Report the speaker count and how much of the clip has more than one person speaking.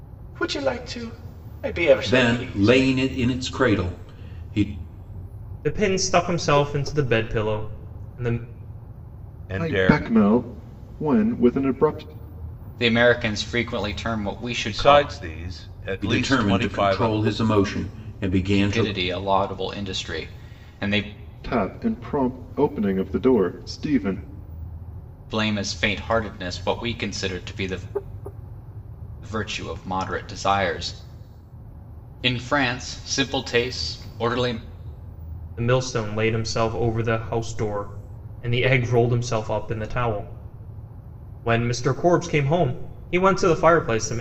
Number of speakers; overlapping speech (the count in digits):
6, about 8%